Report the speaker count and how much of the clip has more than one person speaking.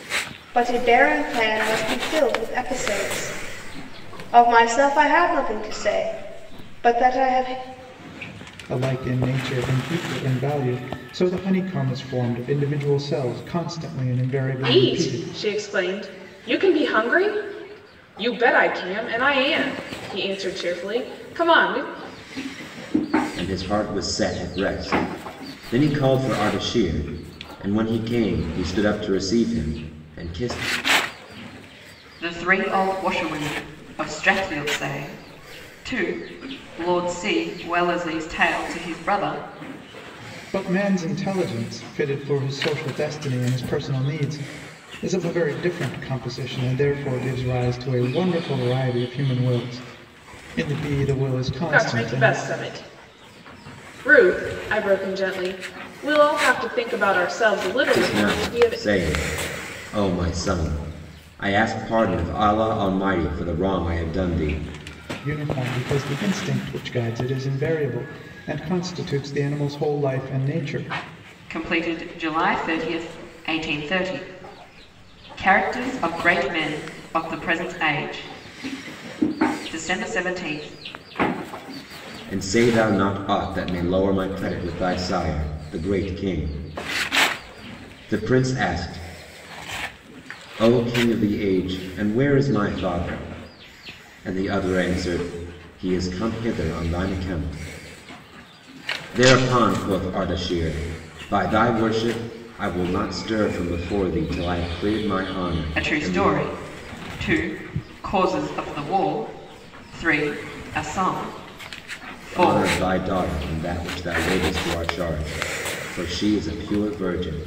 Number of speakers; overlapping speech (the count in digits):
5, about 3%